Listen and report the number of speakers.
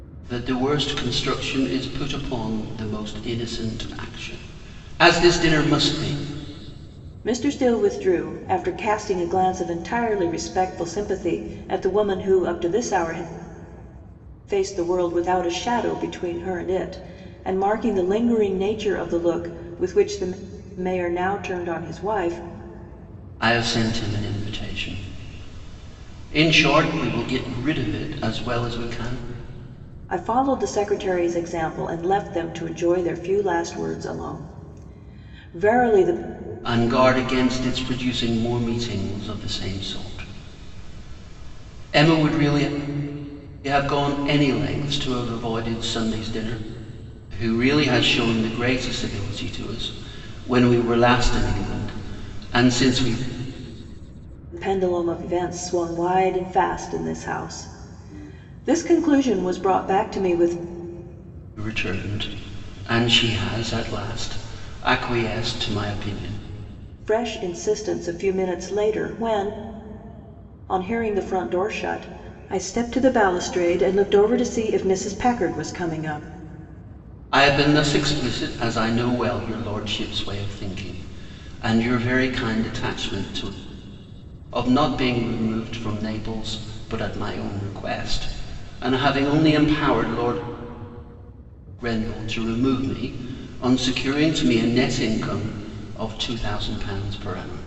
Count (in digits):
2